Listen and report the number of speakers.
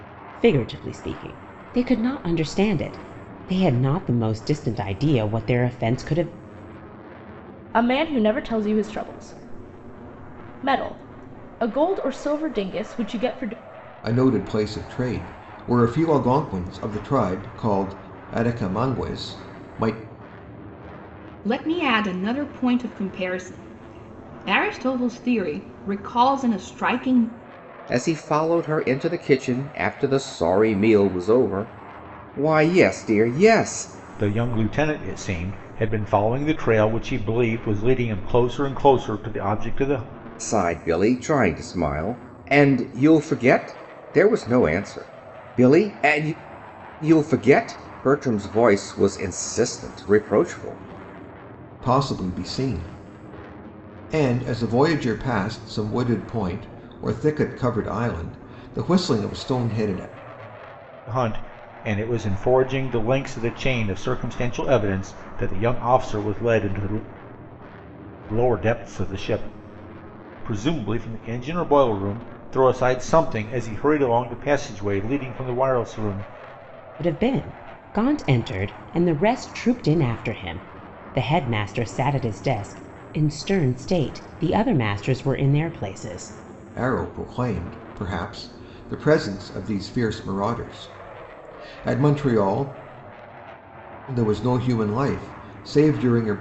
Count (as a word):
six